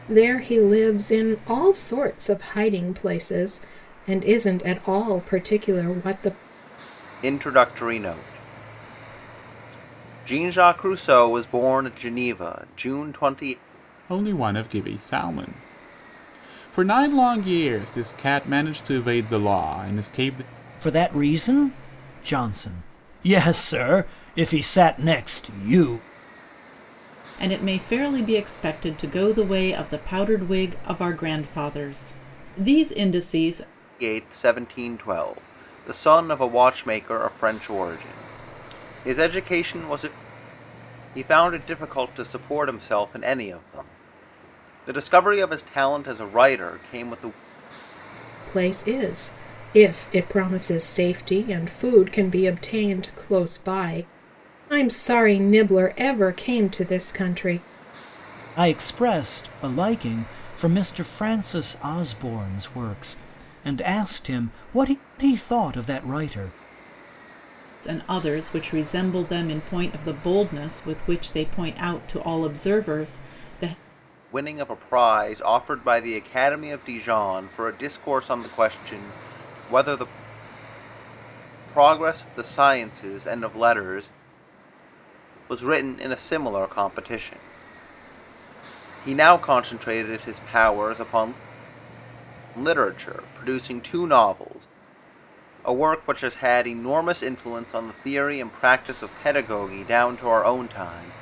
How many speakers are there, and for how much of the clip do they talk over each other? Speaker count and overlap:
five, no overlap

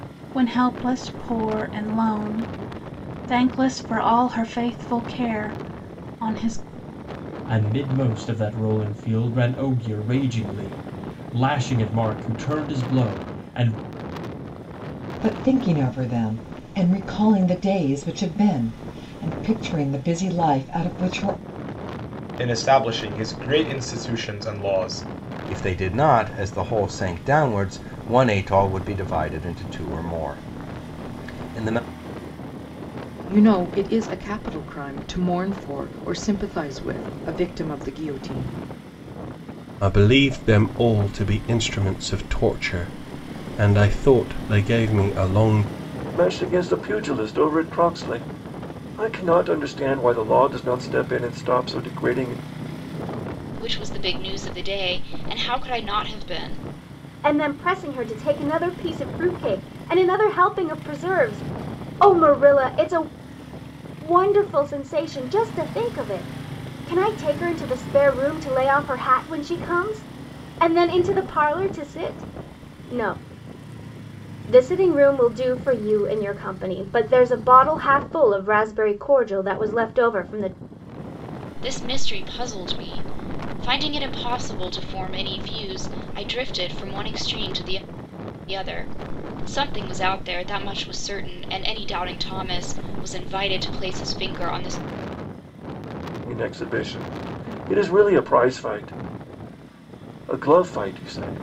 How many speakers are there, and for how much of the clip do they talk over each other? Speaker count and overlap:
ten, no overlap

